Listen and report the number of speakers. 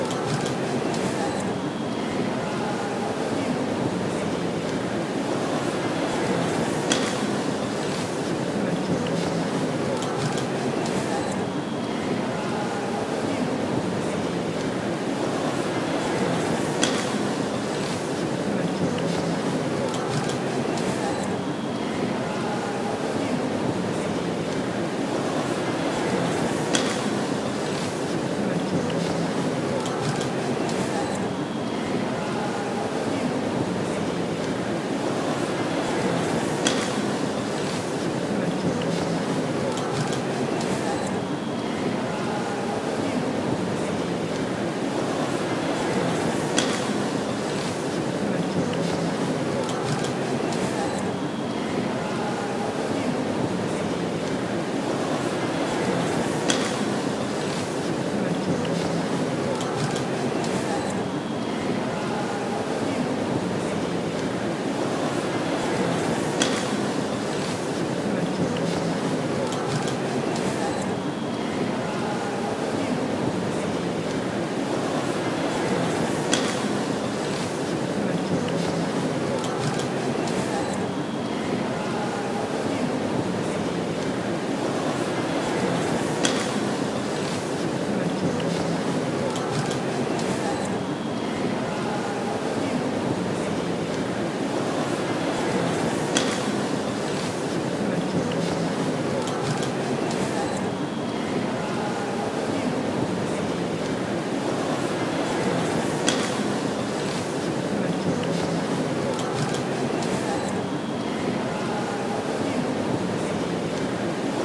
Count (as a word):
zero